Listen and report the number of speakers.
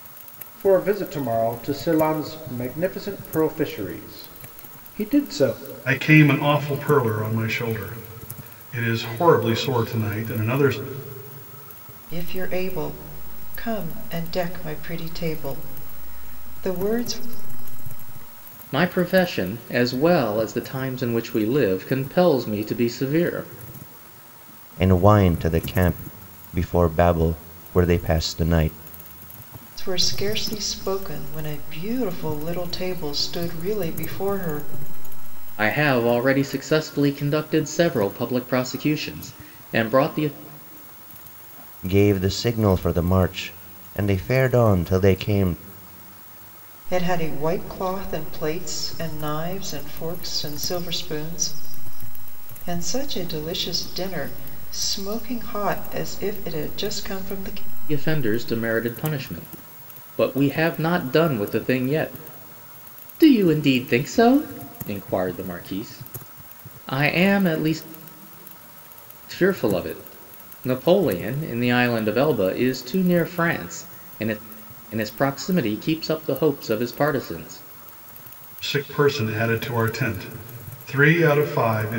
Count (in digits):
5